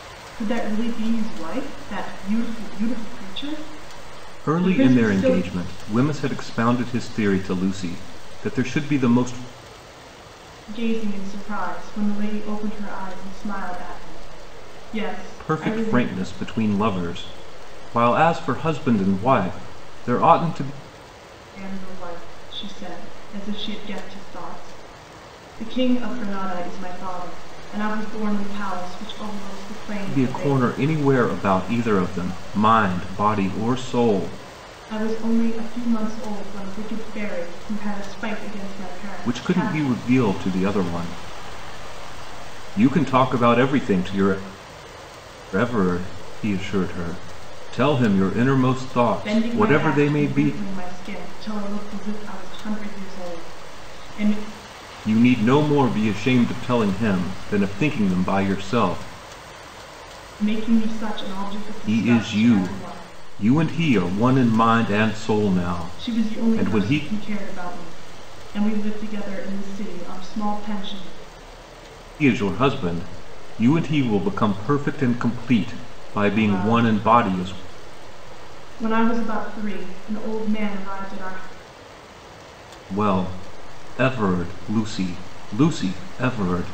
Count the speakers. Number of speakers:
2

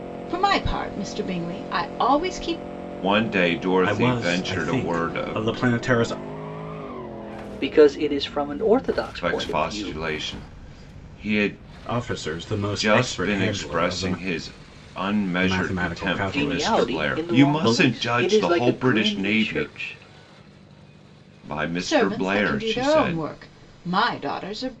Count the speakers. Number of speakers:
4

